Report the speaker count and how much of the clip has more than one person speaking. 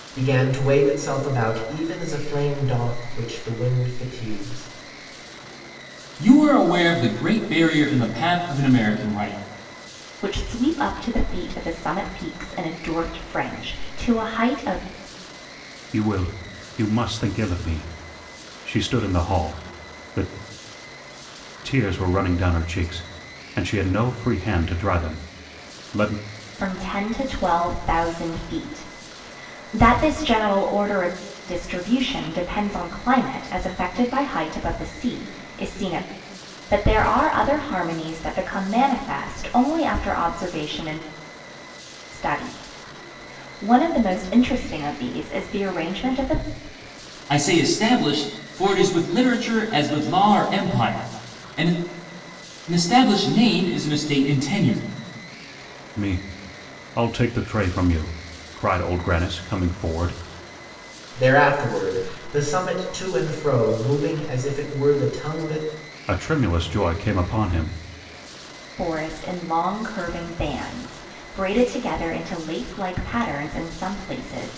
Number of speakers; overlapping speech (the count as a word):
four, no overlap